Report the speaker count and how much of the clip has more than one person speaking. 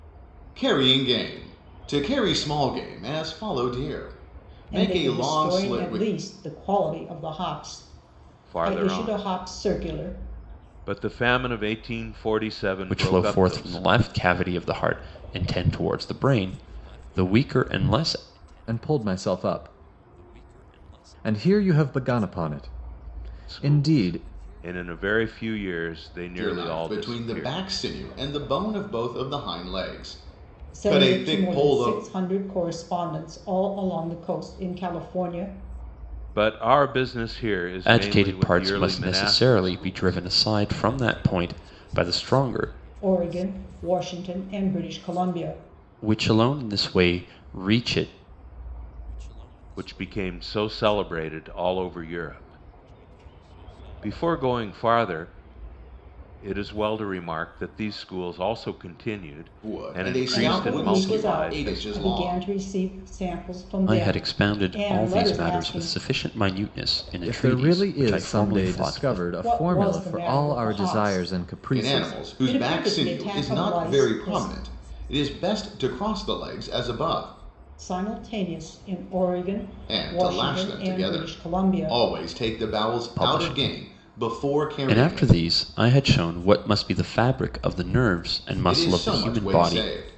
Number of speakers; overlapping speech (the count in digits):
5, about 31%